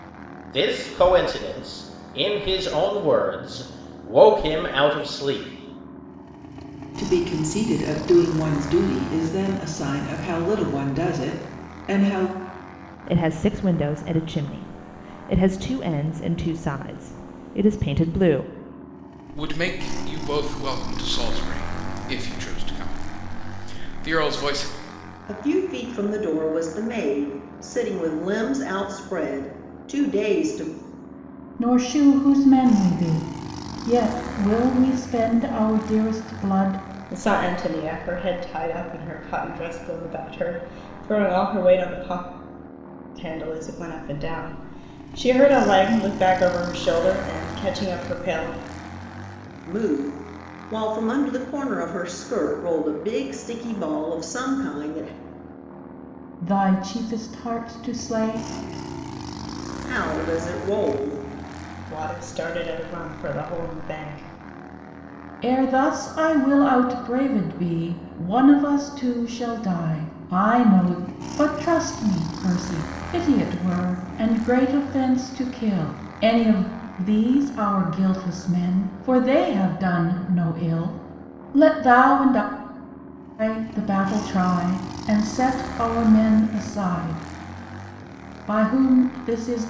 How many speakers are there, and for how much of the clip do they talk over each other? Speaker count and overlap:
7, no overlap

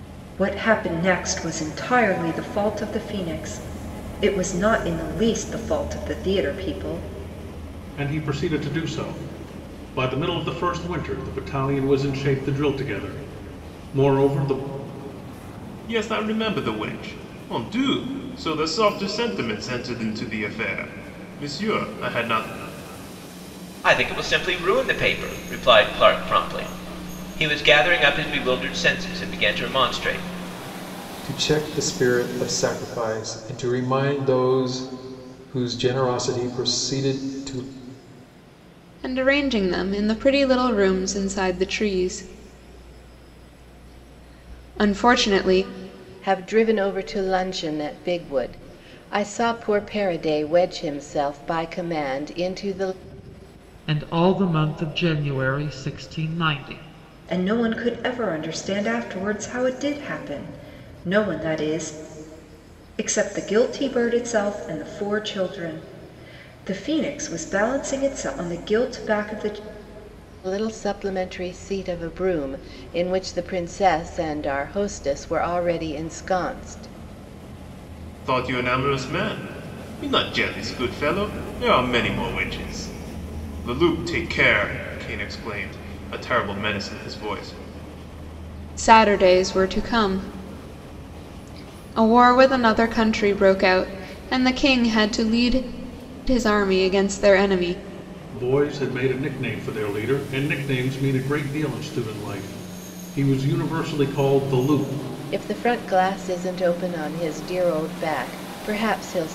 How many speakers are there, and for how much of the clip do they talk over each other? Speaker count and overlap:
8, no overlap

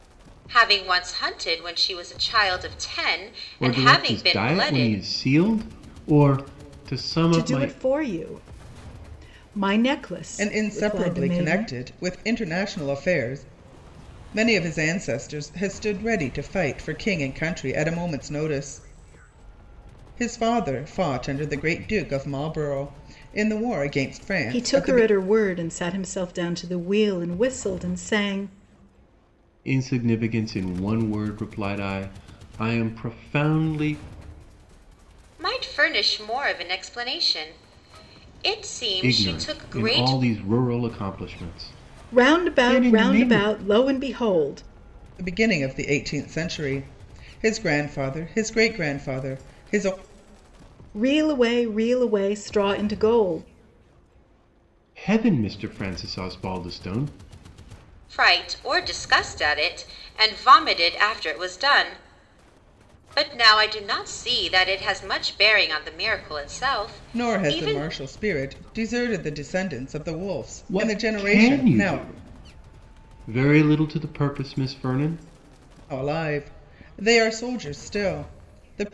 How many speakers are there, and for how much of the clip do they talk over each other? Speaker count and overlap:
4, about 11%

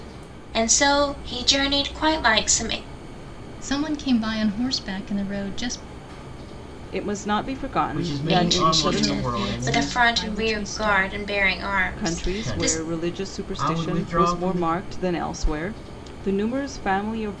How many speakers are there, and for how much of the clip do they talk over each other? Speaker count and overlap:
4, about 35%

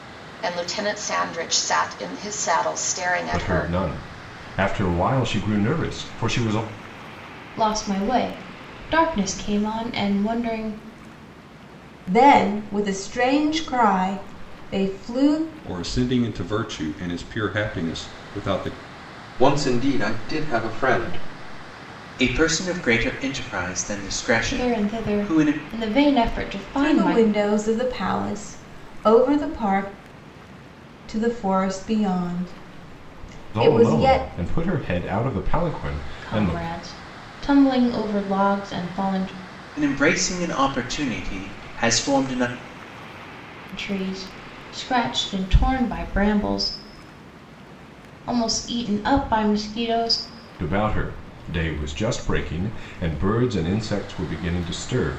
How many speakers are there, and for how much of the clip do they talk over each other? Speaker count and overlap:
7, about 6%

